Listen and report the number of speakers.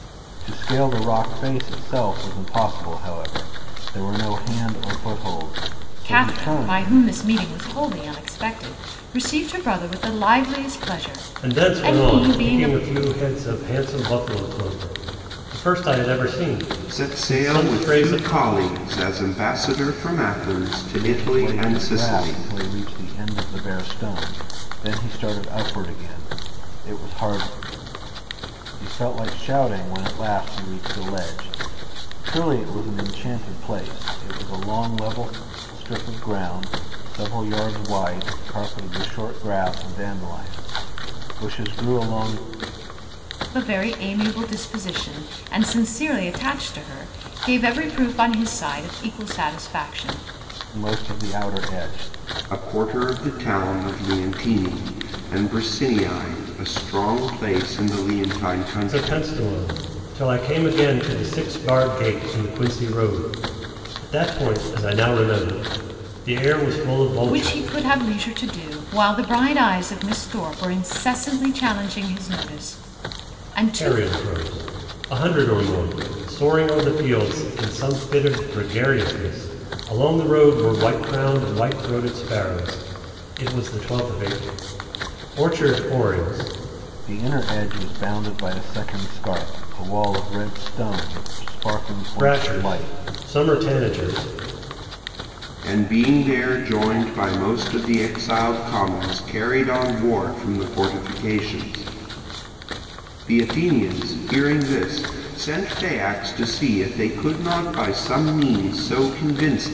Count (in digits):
4